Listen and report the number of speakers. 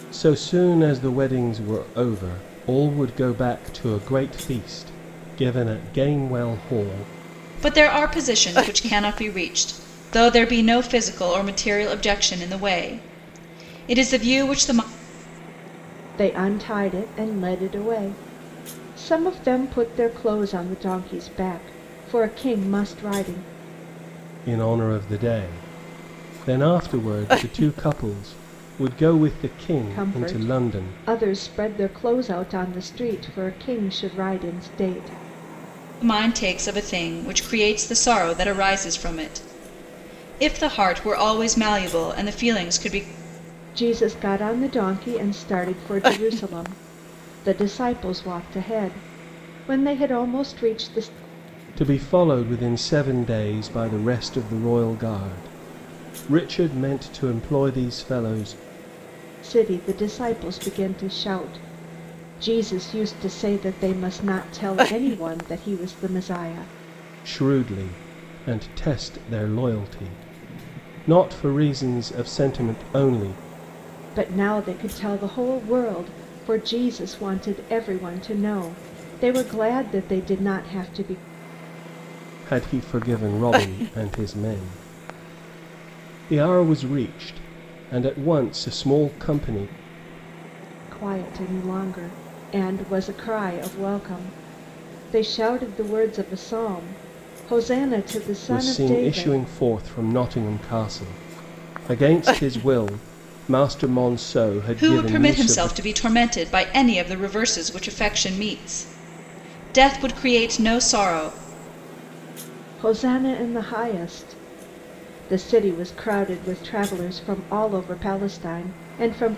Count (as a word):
three